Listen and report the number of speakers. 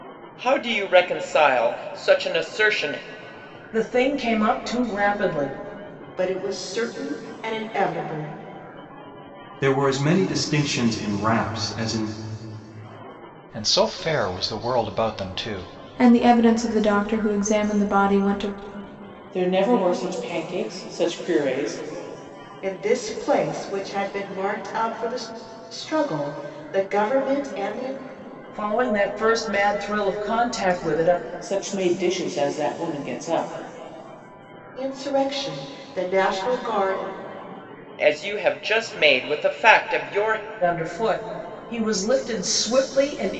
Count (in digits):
7